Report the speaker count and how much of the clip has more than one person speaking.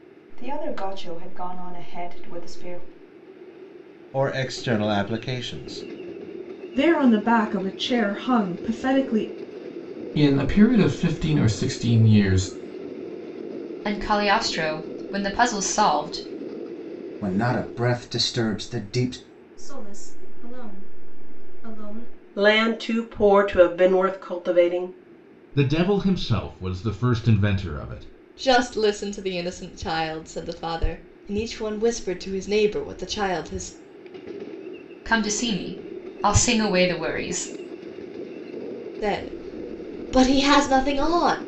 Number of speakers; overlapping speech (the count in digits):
10, no overlap